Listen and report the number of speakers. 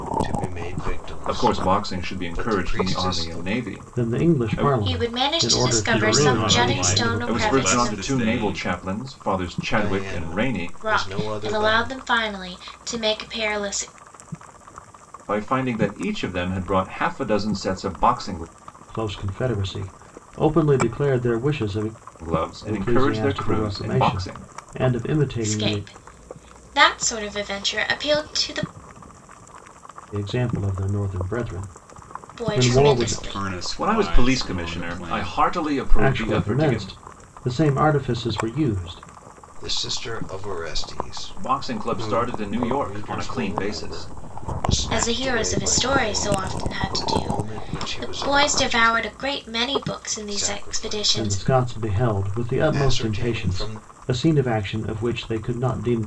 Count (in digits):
5